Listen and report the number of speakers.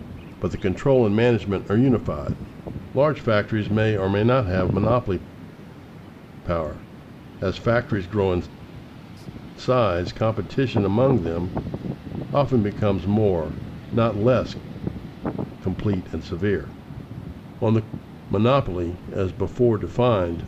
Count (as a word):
one